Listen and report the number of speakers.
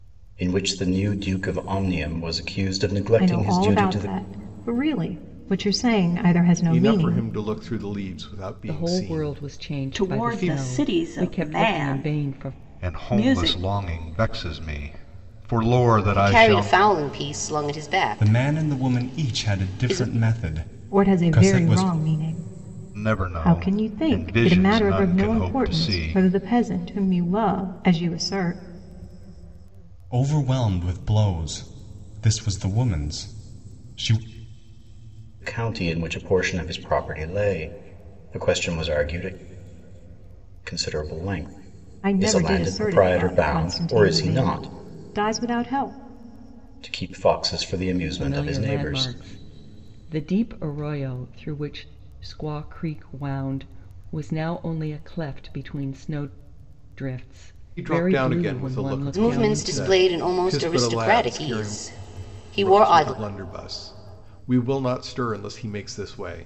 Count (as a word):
eight